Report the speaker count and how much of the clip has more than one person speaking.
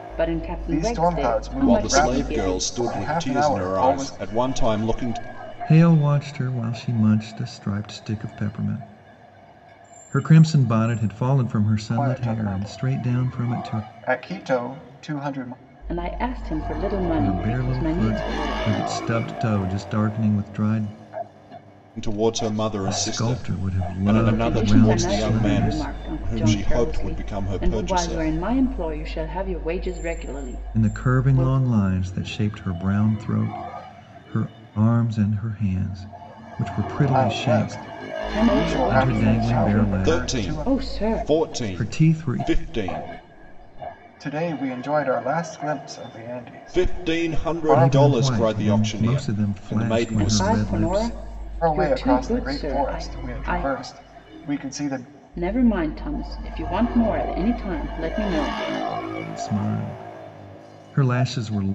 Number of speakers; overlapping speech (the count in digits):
4, about 41%